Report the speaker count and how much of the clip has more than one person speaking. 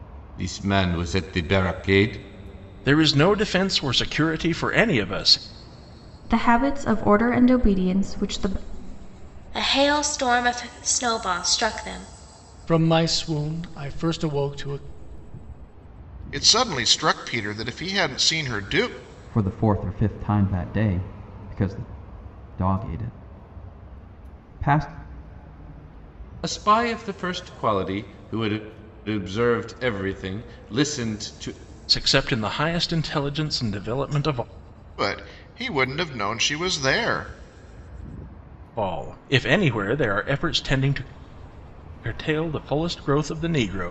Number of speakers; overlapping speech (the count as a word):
seven, no overlap